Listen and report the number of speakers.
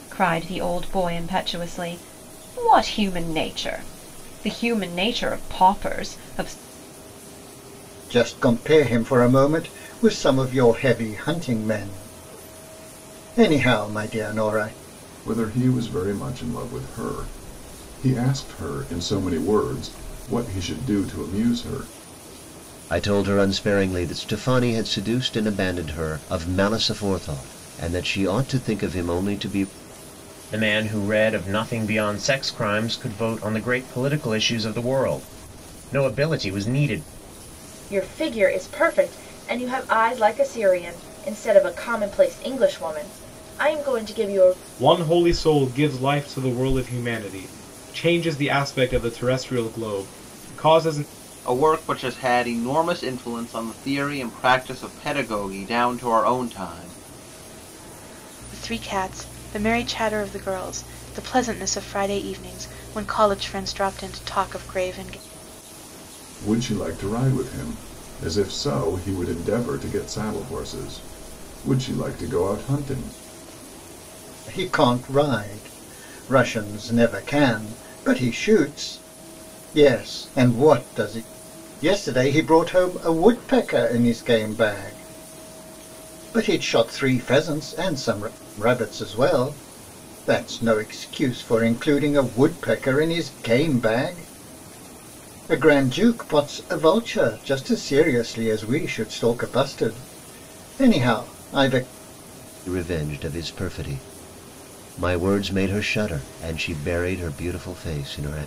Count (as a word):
nine